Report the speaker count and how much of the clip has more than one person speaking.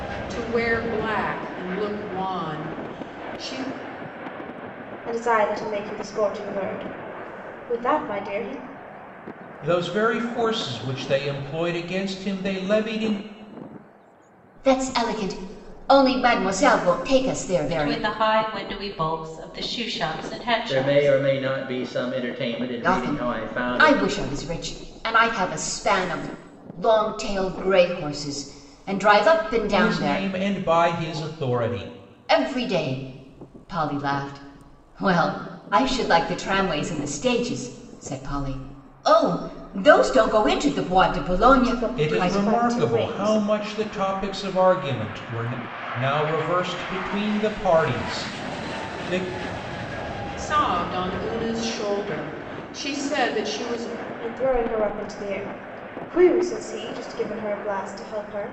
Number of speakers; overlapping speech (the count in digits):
6, about 8%